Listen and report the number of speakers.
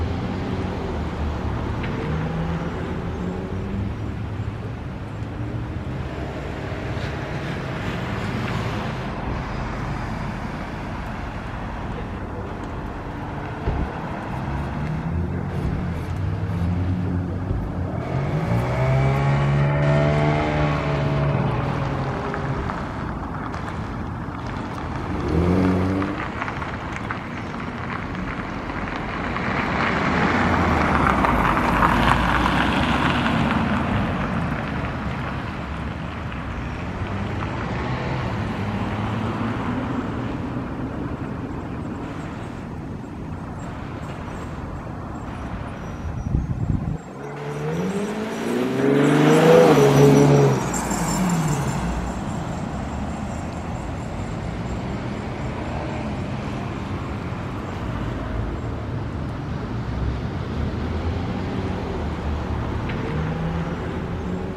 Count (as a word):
zero